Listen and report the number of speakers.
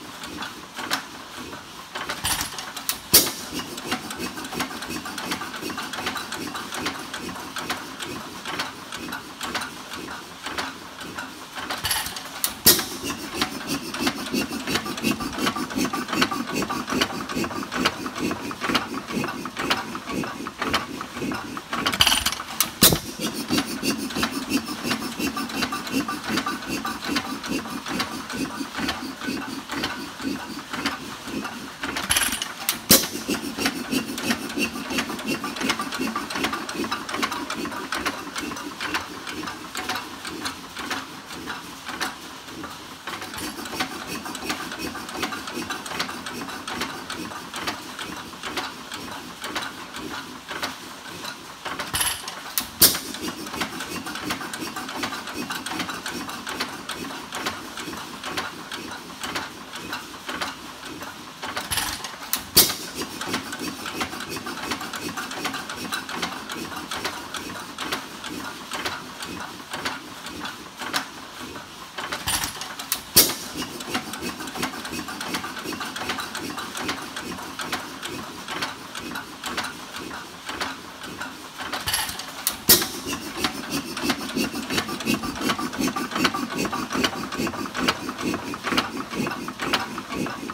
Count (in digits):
0